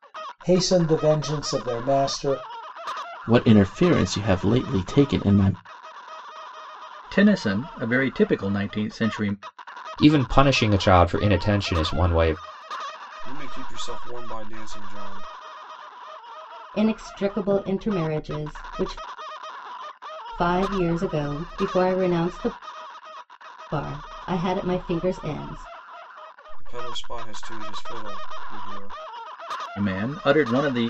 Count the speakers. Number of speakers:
6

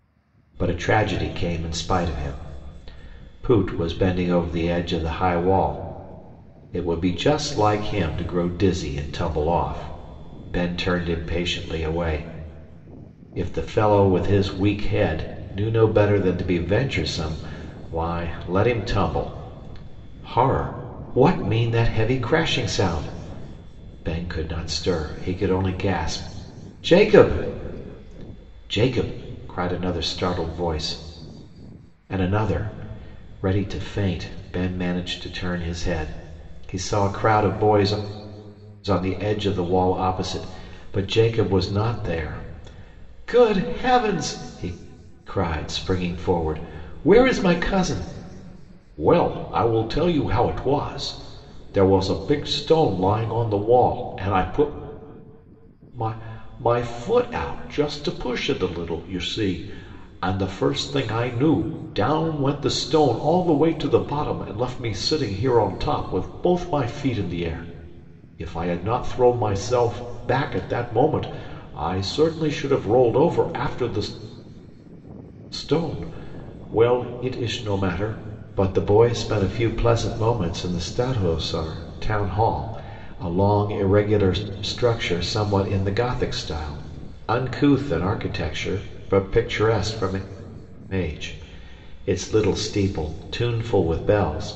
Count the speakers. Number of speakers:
1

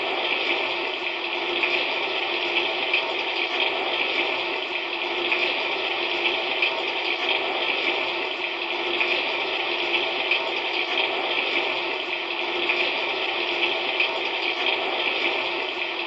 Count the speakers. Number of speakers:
0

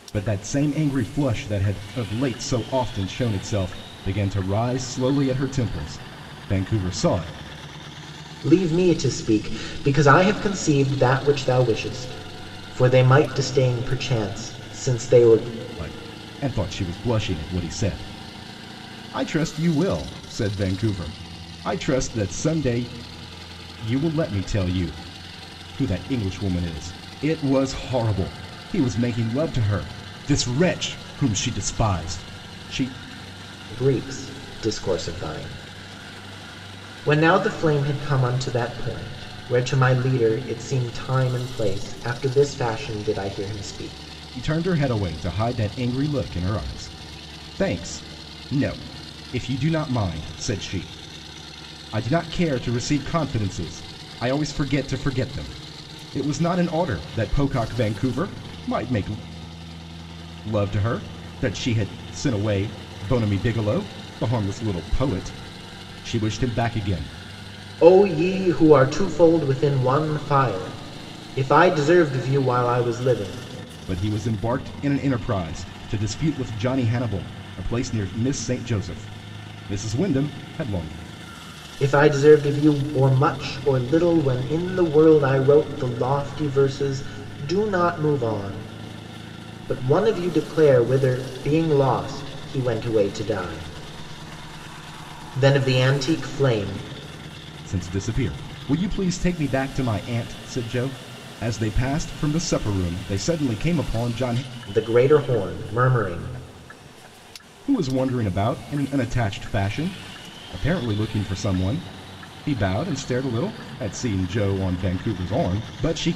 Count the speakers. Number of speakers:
2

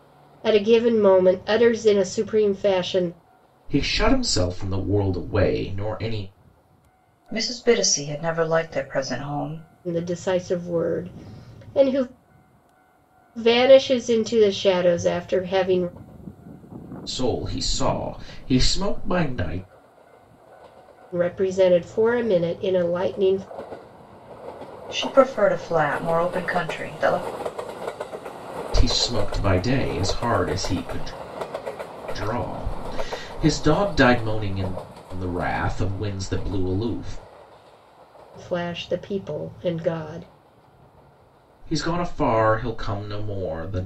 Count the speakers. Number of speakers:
3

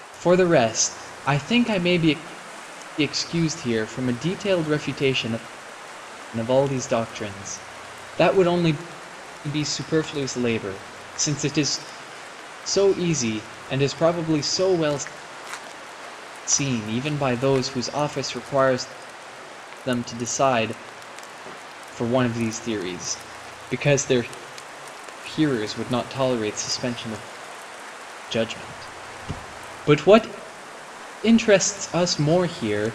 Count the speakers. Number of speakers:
1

